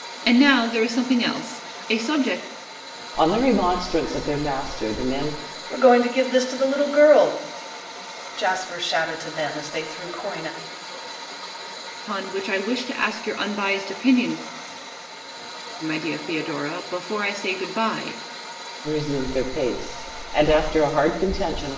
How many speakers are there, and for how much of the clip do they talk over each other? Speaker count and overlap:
three, no overlap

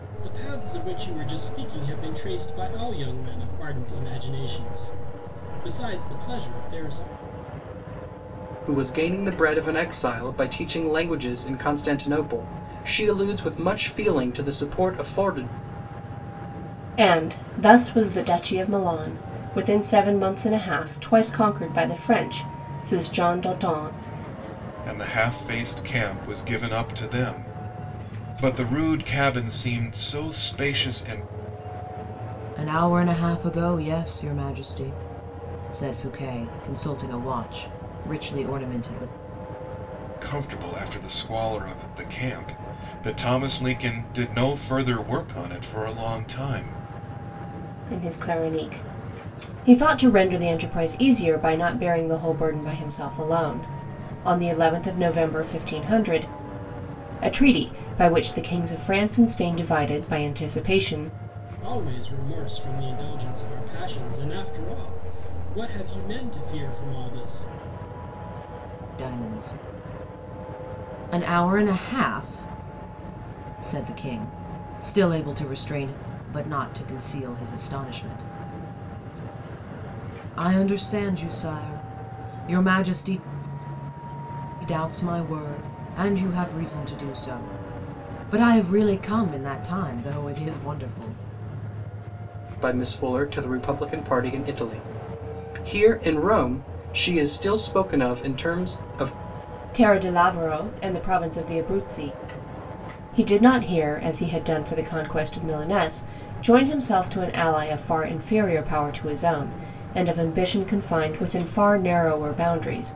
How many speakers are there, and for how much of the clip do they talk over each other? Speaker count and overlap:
five, no overlap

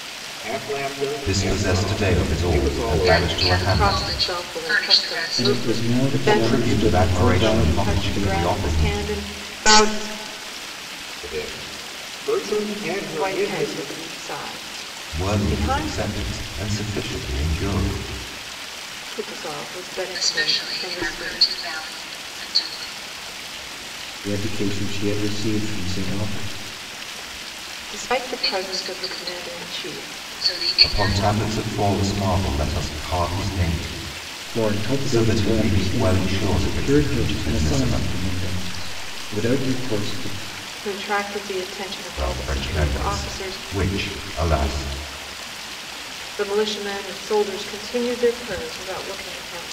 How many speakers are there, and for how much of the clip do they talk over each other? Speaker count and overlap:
five, about 35%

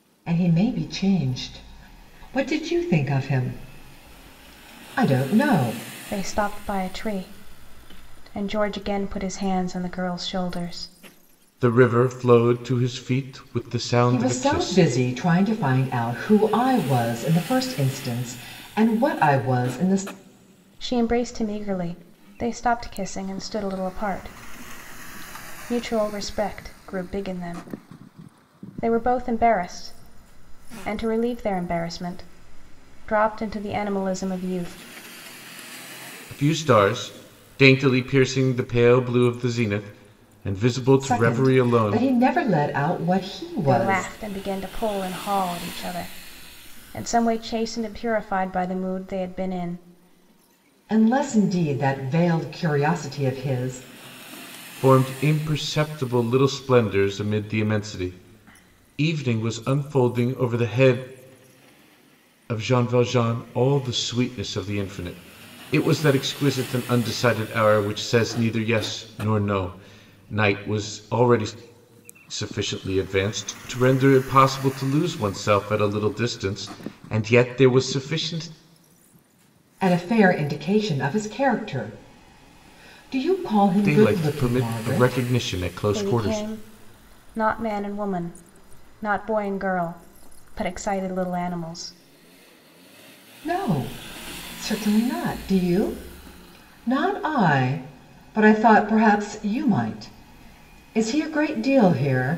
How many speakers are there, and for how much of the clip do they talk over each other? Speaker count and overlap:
three, about 4%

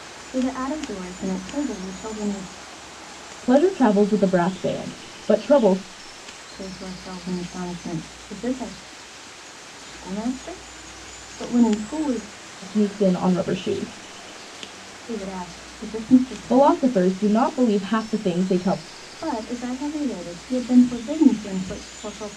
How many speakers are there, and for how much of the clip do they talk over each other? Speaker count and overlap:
two, about 2%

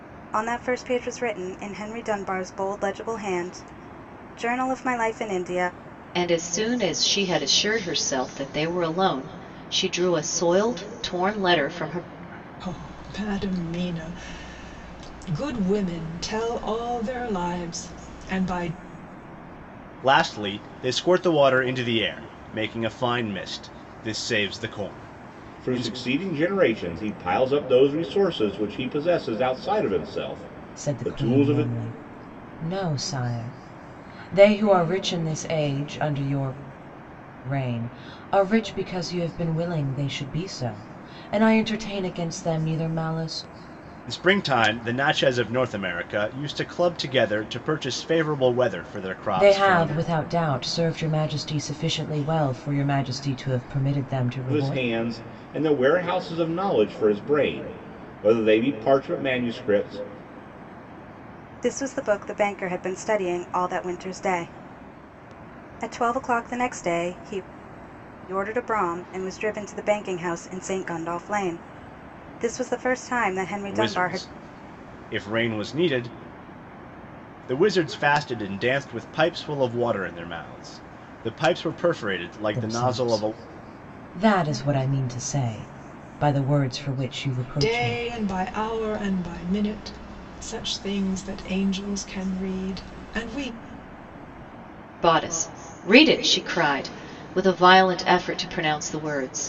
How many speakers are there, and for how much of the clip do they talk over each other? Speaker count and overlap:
six, about 4%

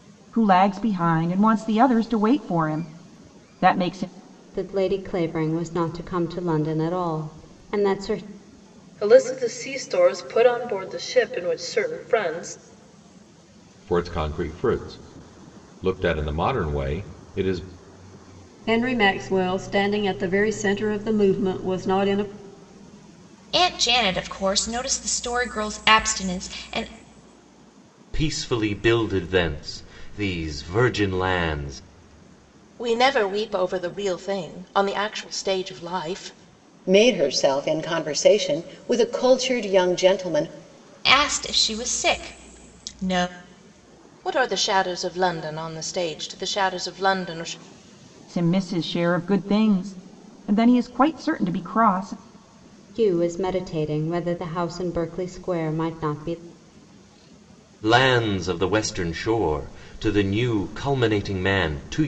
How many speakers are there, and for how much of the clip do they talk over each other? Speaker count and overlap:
nine, no overlap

